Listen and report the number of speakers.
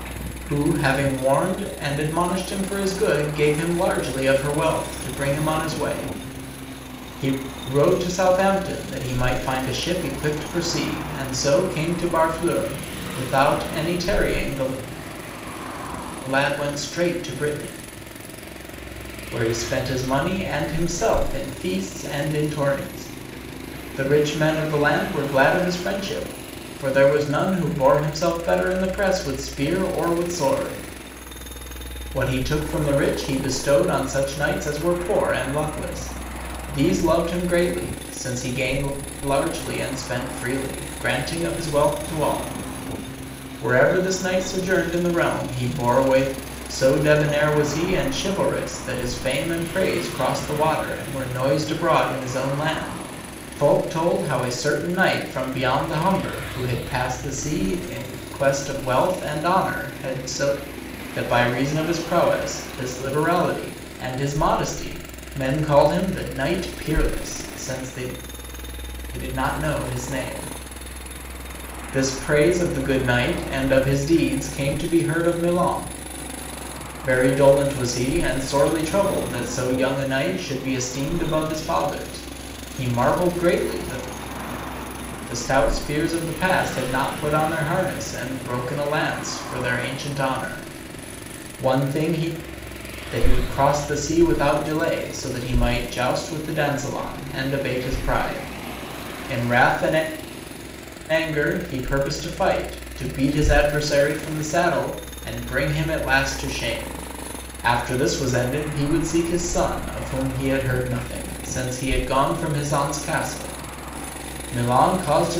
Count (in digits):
1